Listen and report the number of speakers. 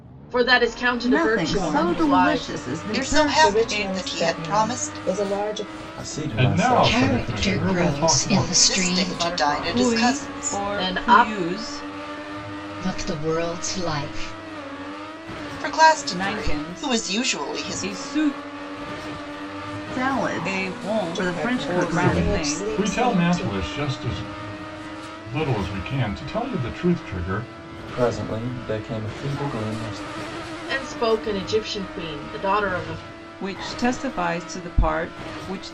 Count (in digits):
8